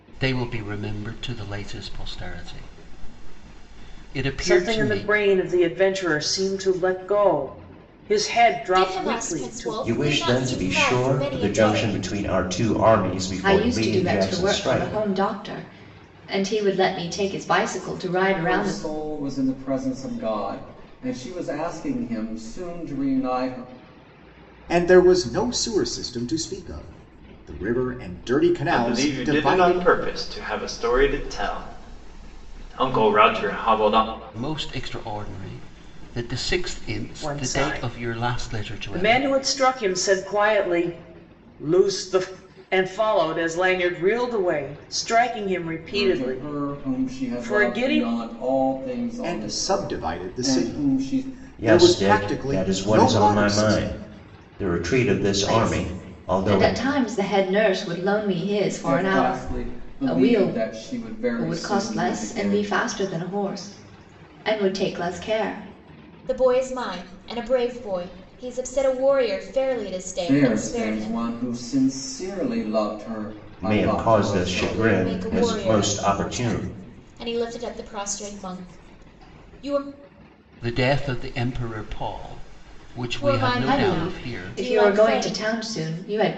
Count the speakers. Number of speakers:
8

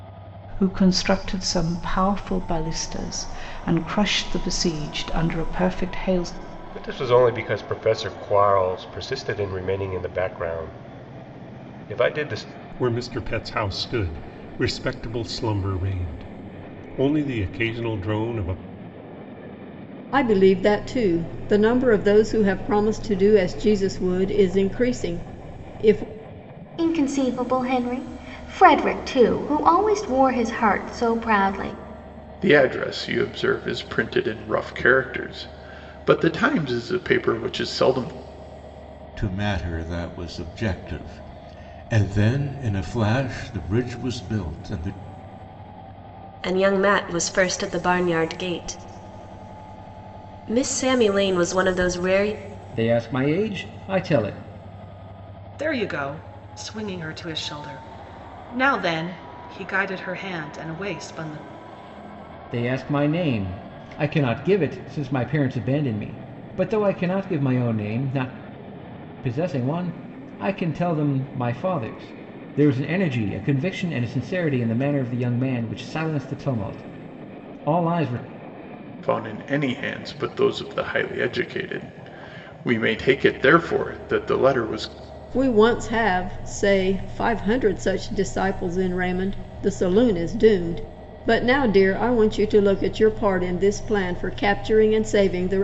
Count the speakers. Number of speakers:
10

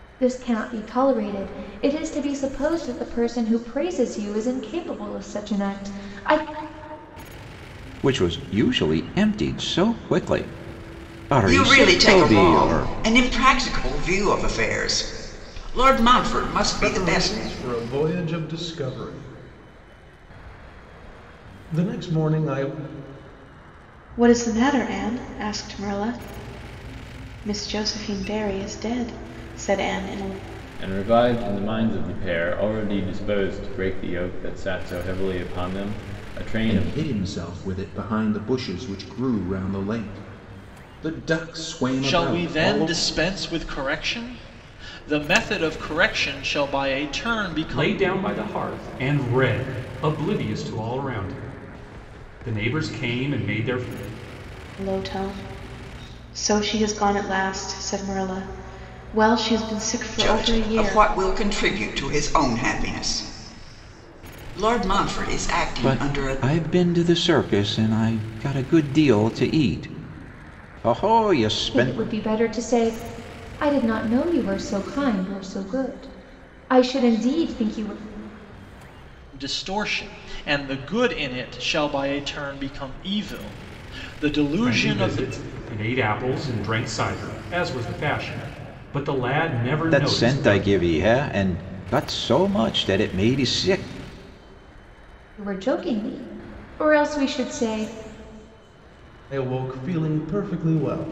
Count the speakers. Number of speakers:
9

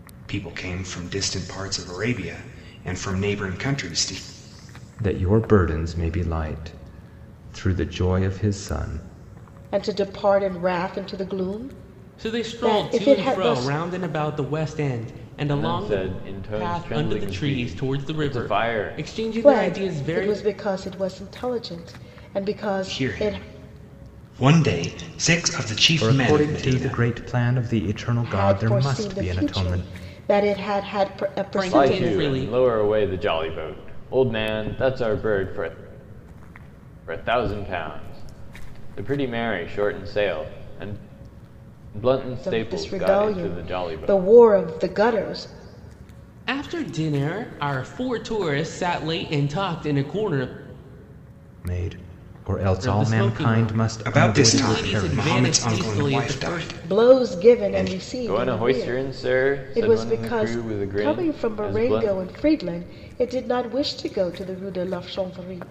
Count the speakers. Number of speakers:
5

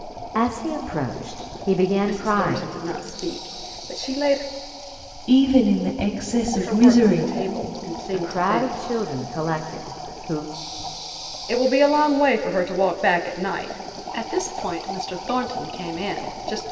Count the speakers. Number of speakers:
3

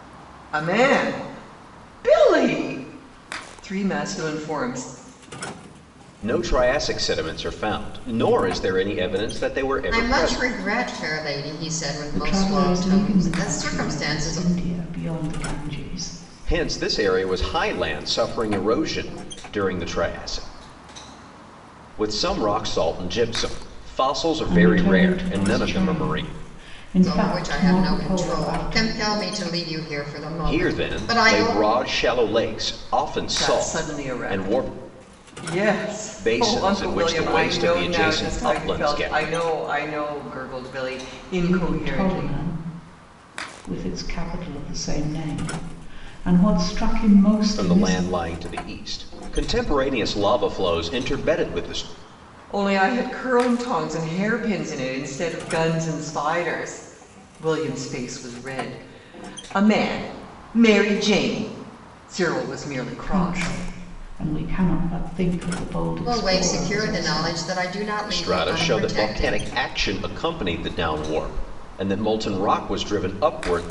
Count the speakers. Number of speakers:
4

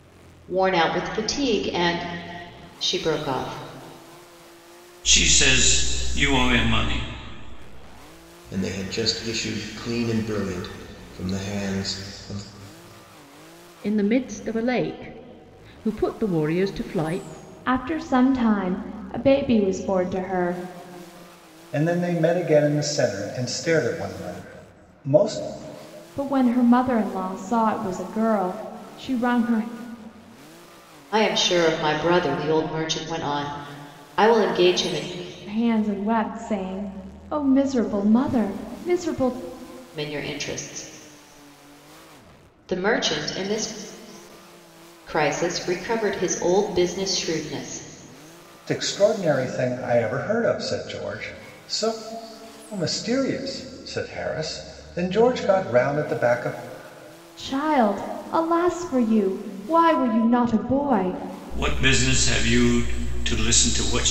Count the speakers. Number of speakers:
6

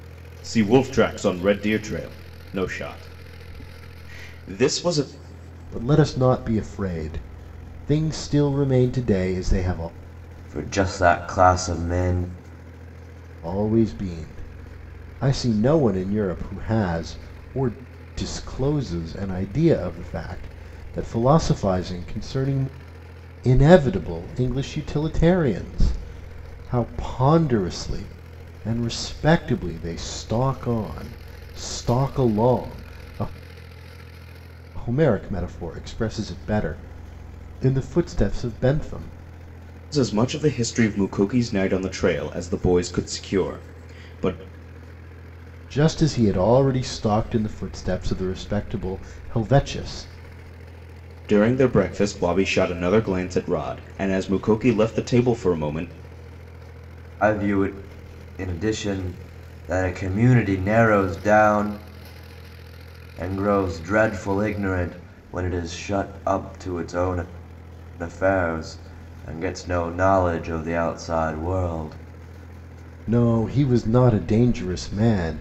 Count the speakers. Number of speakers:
3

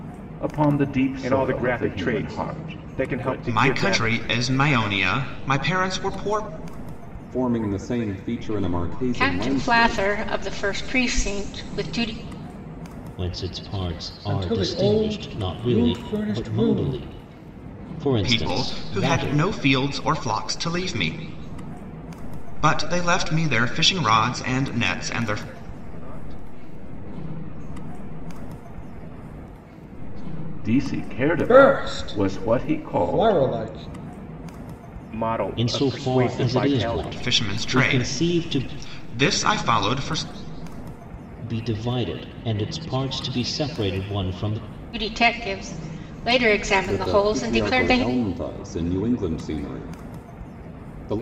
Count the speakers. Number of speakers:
8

